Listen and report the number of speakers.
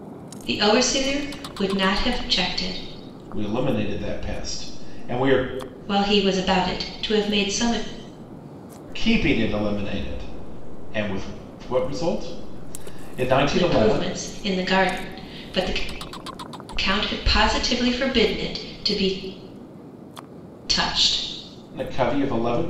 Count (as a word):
two